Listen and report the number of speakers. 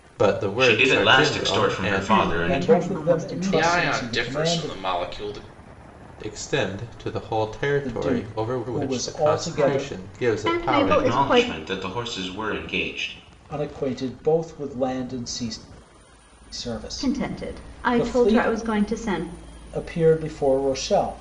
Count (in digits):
5